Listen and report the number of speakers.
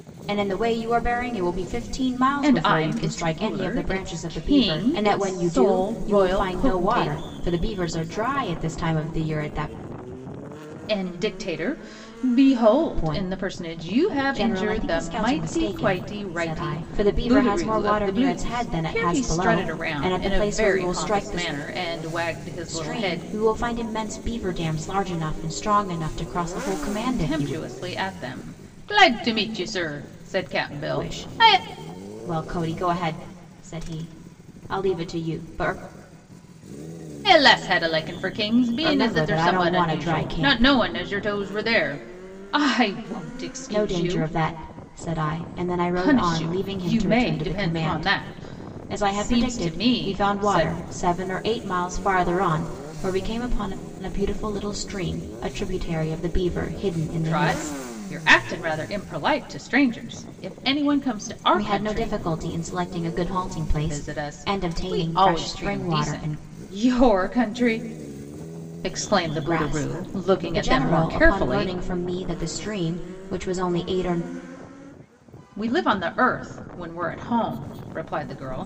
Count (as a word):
two